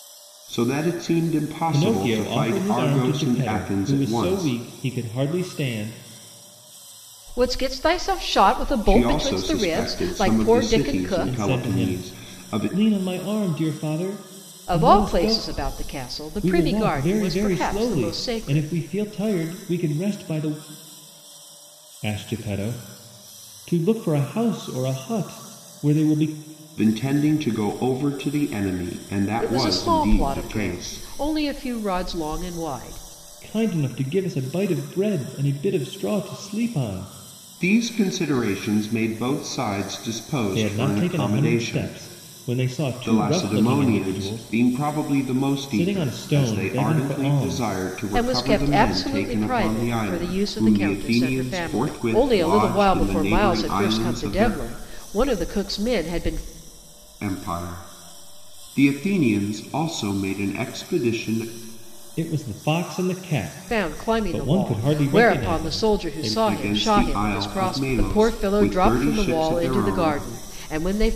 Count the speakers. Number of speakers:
three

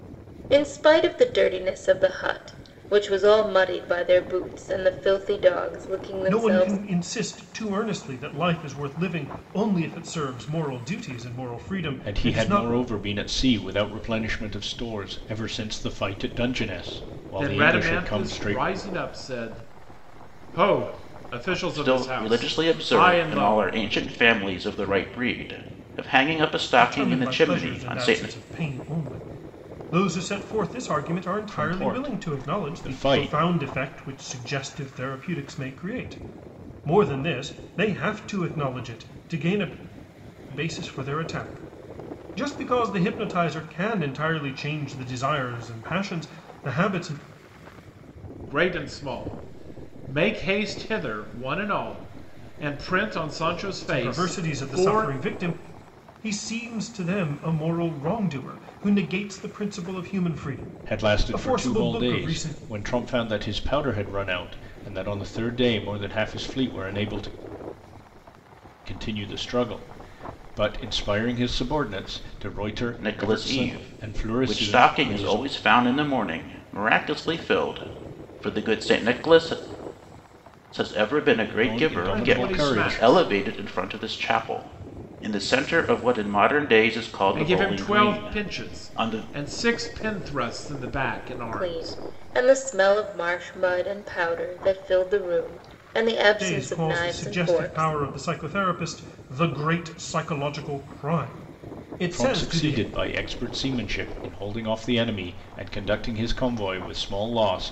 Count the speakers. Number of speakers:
five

